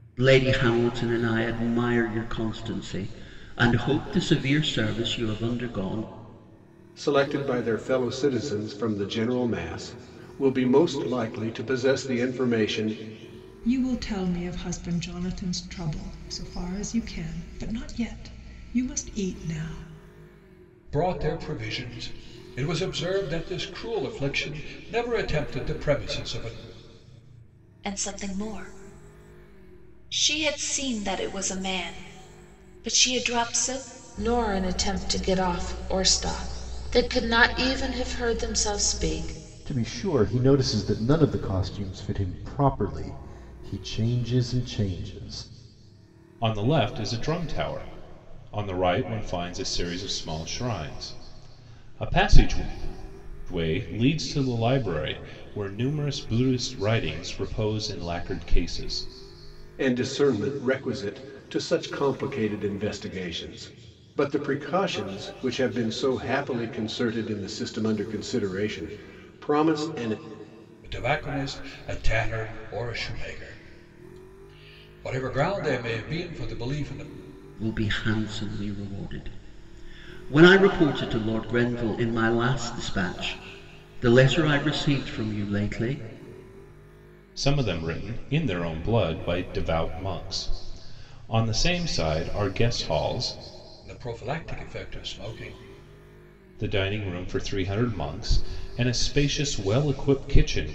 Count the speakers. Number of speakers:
eight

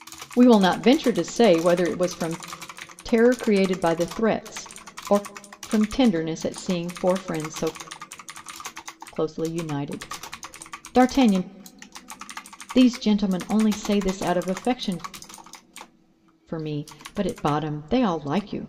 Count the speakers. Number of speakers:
one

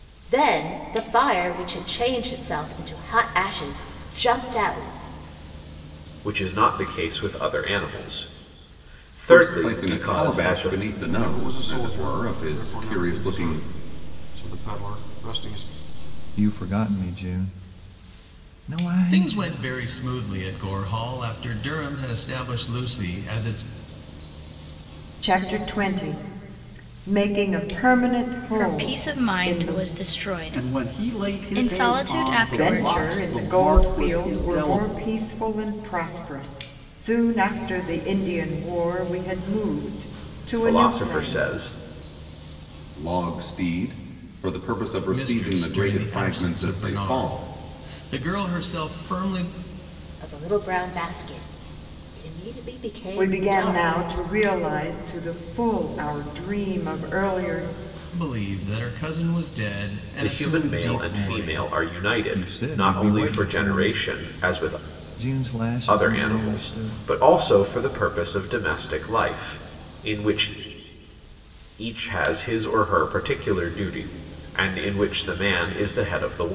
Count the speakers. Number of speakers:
nine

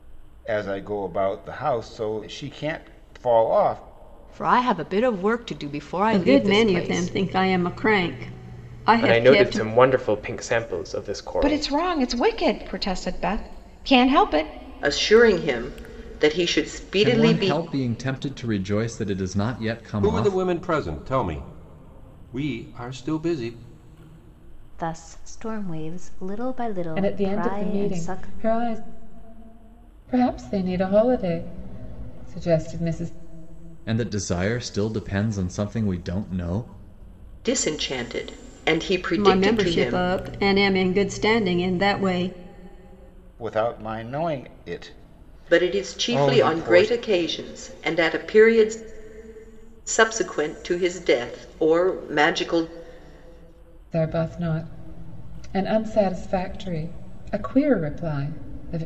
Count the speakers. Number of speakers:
ten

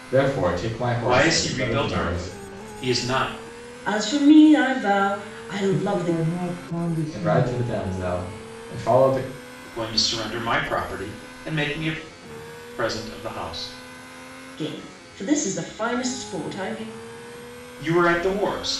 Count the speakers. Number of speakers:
four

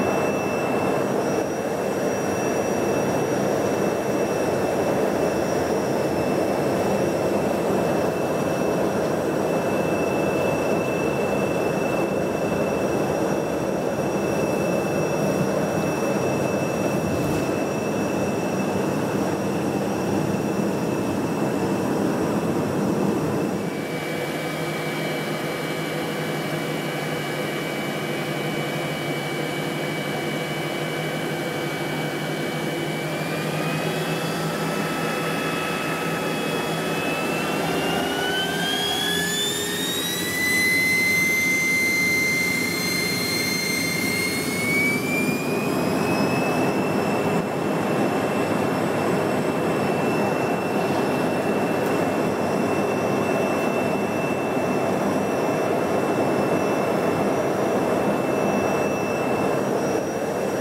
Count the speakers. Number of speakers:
zero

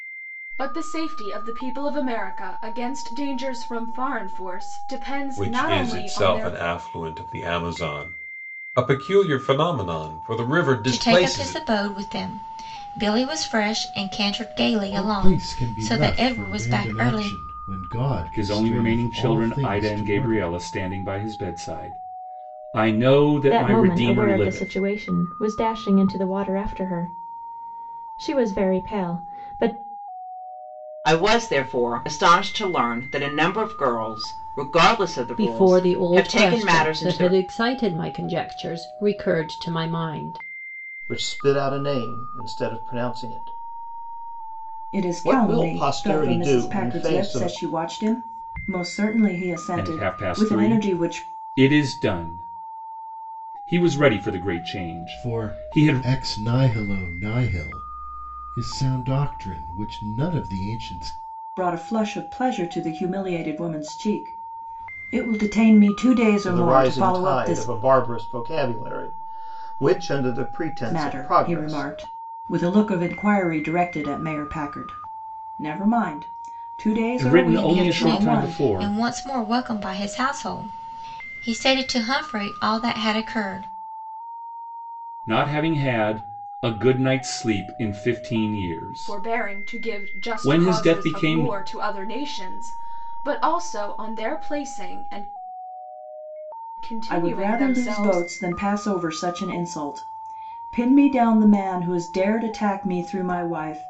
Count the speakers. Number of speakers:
ten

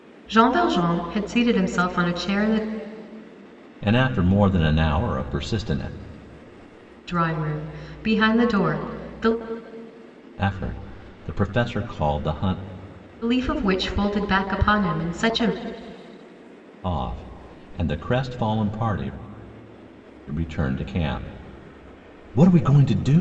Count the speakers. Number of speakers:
two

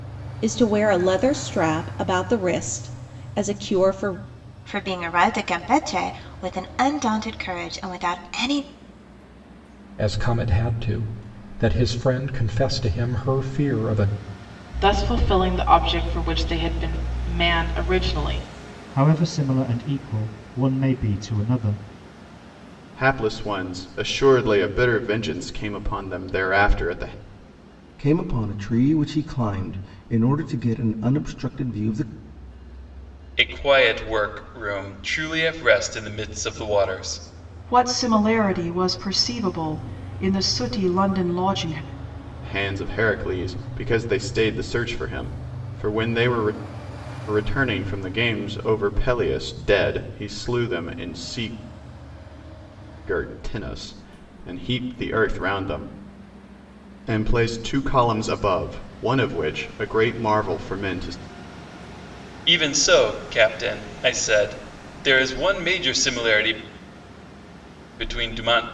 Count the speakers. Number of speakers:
nine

